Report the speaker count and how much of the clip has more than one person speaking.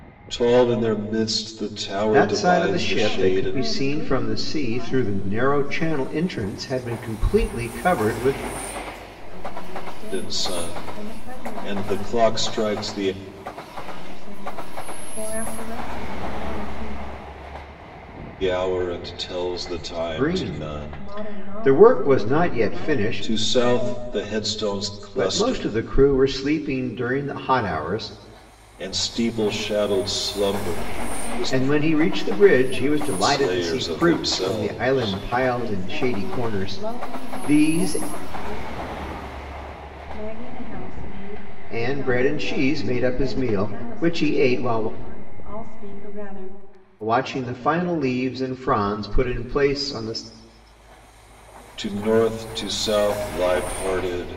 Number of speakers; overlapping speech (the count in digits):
3, about 39%